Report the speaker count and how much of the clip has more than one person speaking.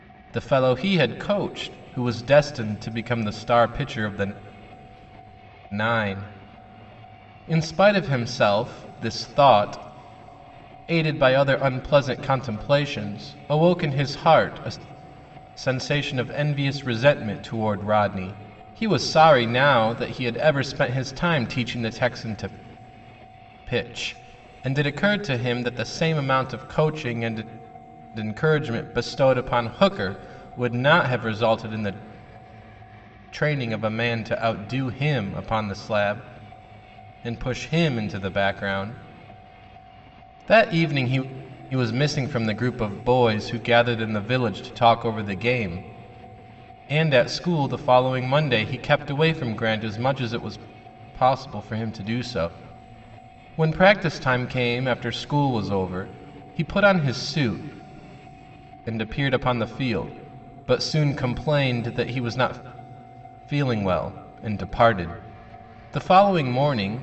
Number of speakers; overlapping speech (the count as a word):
one, no overlap